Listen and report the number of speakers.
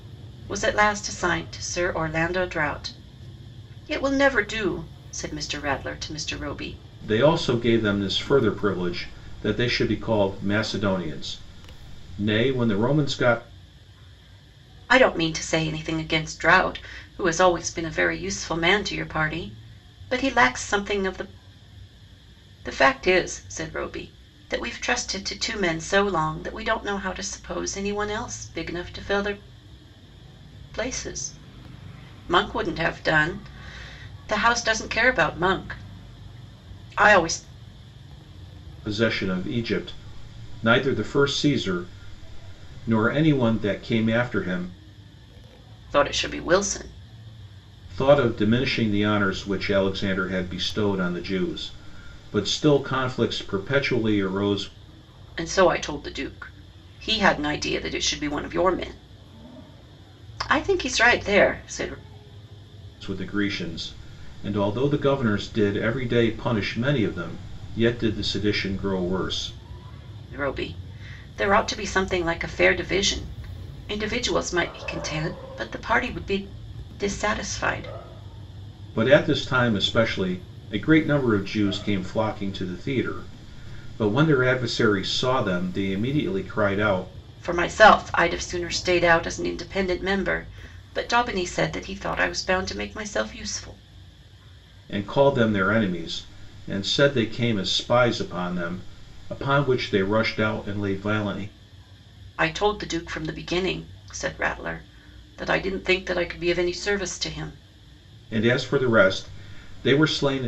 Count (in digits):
2